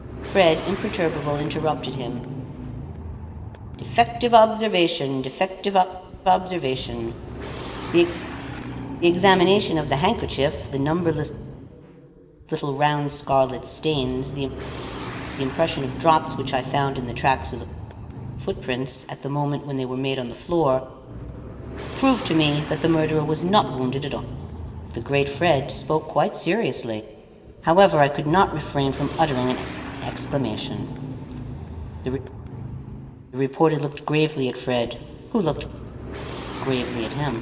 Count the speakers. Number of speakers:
1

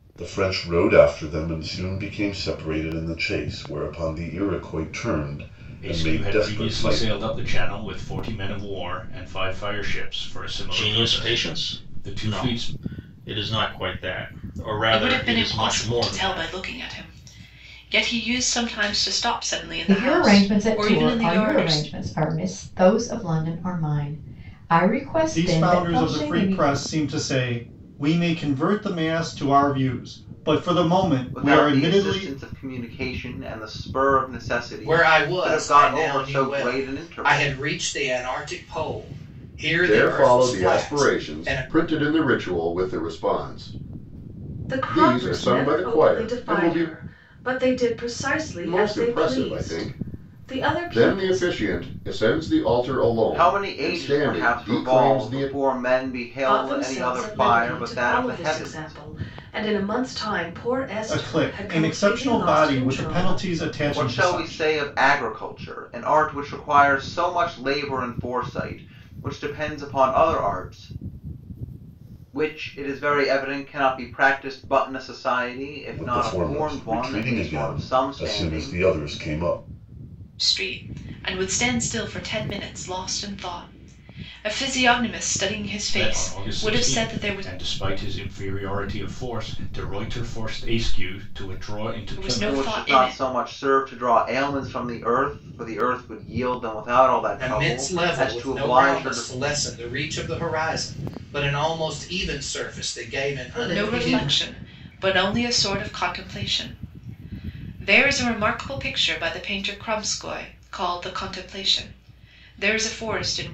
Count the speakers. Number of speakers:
10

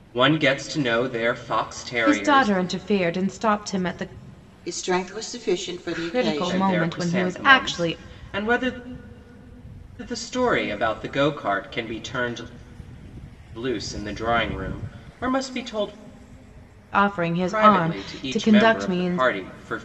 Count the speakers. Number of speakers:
3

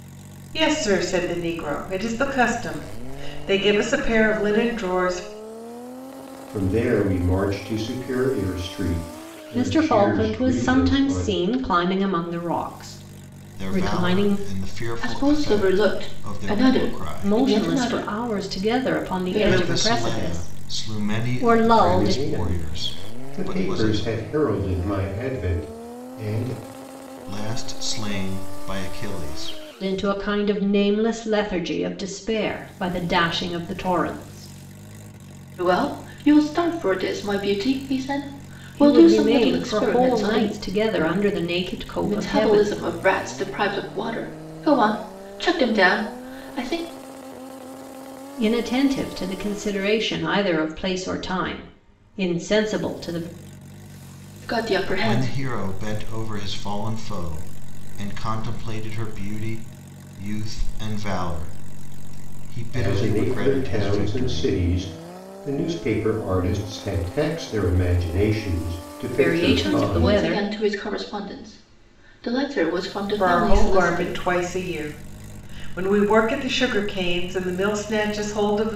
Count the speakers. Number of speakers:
5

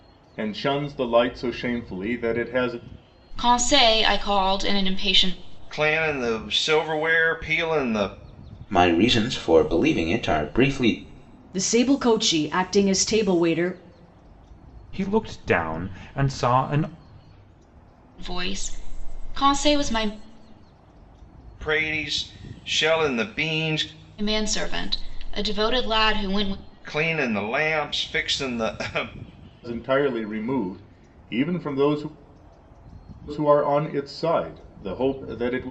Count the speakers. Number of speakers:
6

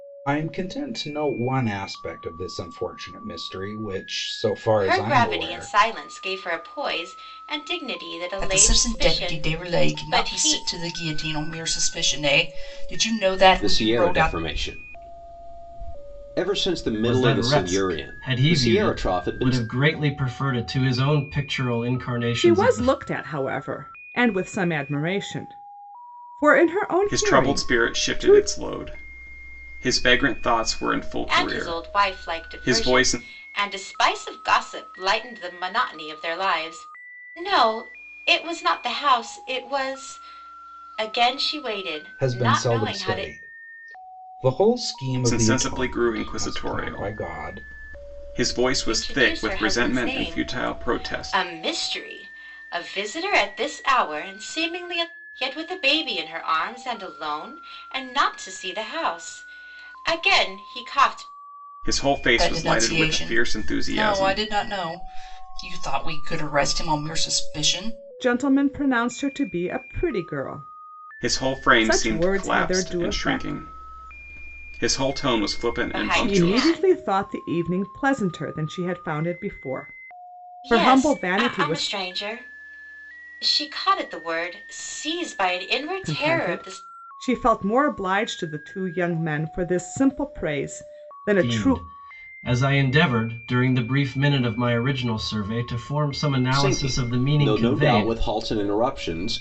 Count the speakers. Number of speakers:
7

